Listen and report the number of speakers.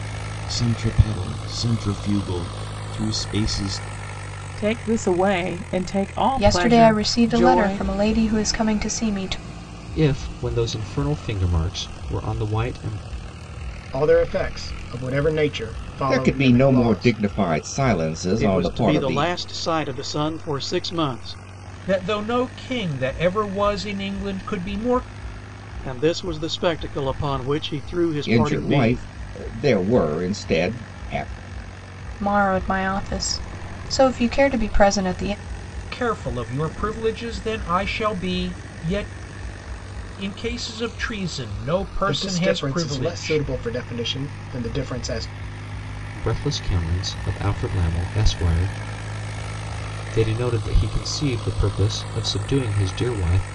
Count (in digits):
8